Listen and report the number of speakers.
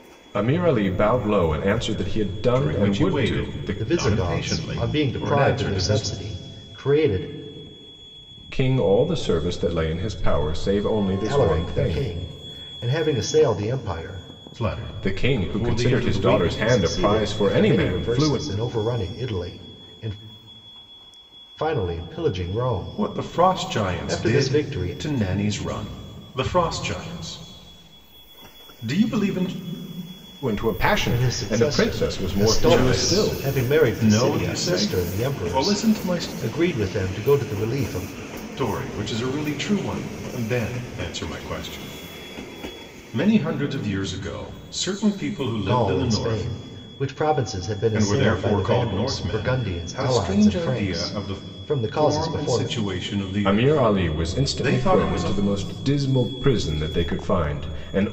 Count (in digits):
3